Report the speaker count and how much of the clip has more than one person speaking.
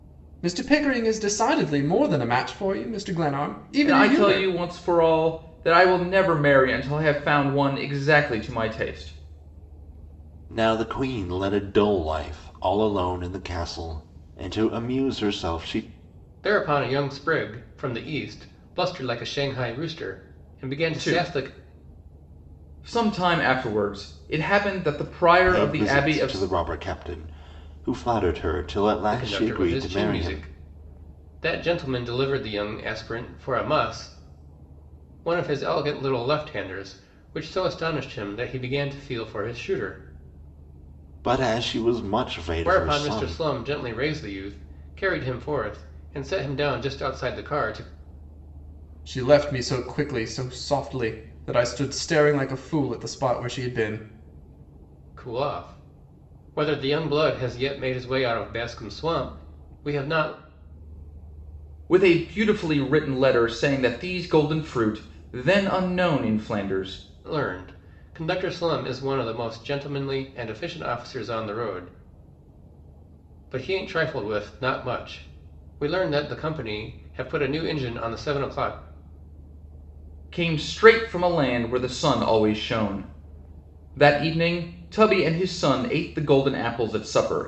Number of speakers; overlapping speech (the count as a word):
four, about 5%